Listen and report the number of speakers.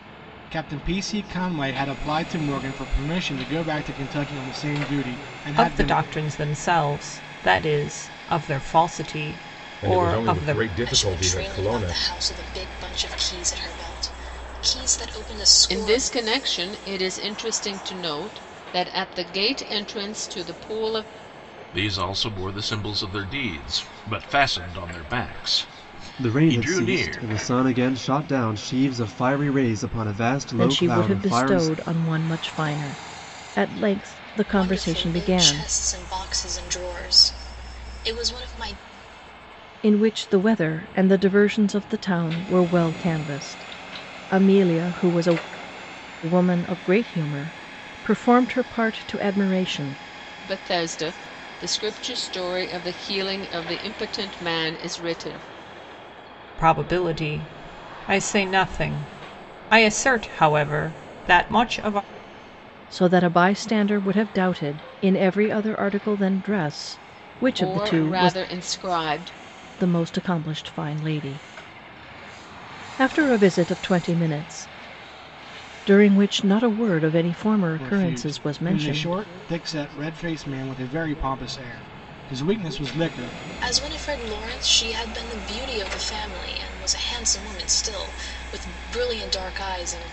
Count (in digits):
8